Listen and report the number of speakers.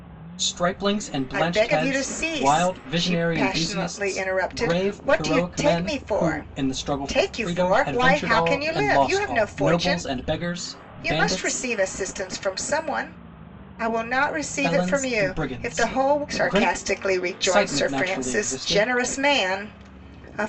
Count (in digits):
2